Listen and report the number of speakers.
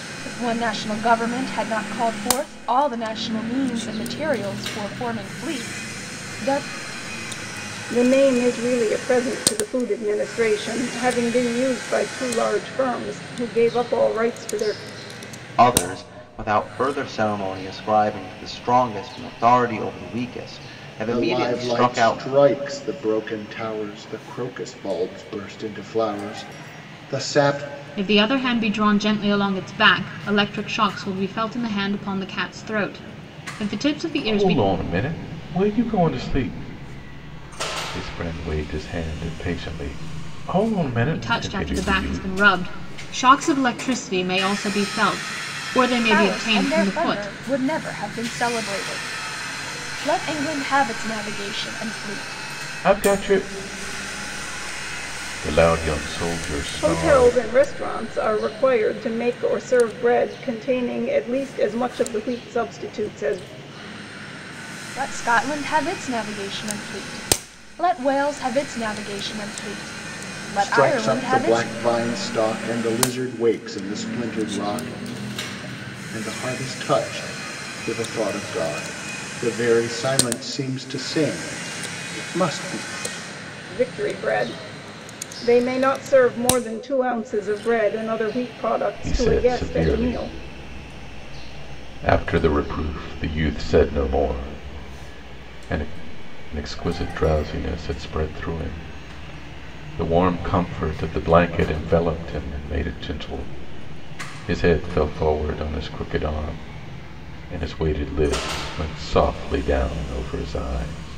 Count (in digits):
6